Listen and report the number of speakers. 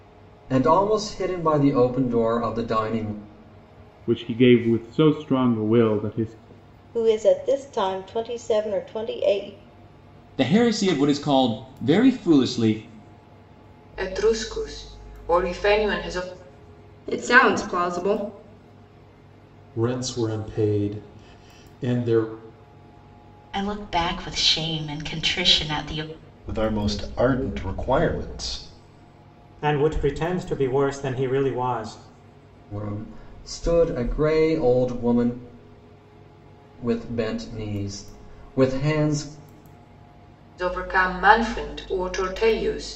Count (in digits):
10